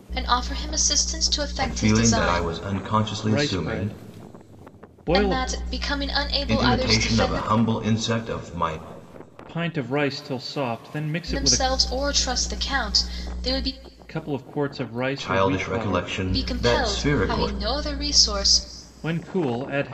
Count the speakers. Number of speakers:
3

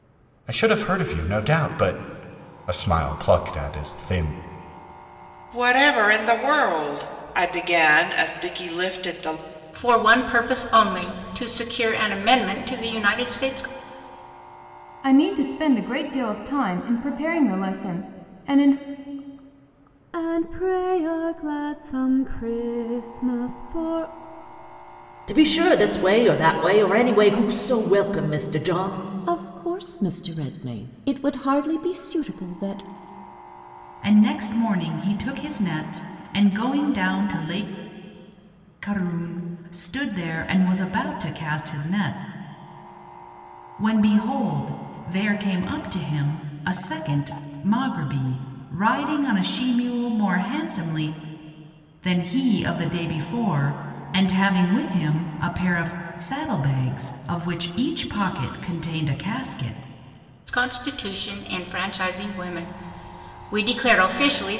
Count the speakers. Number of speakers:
8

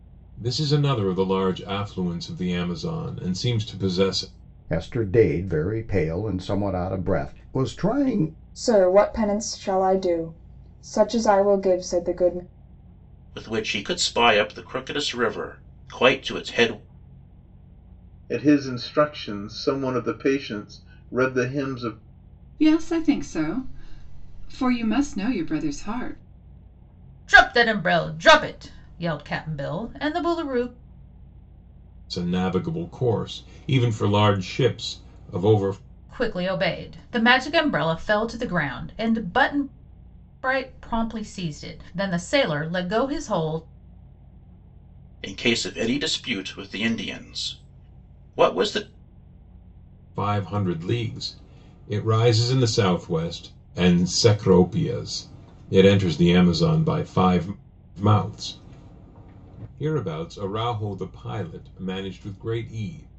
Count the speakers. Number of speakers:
7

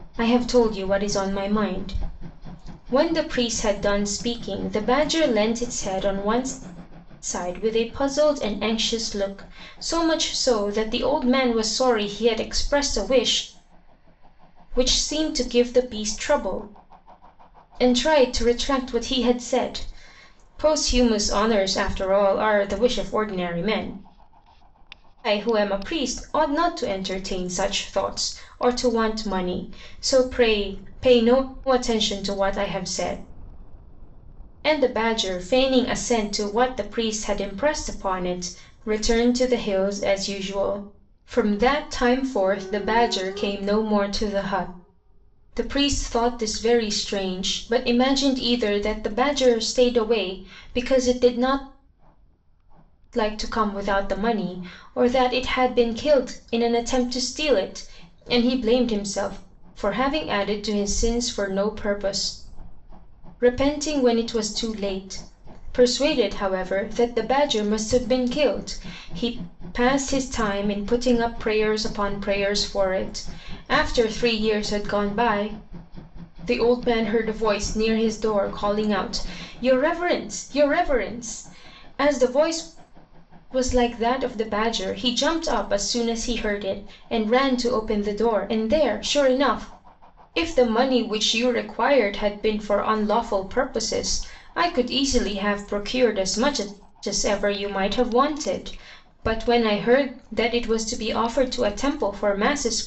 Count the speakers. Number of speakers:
1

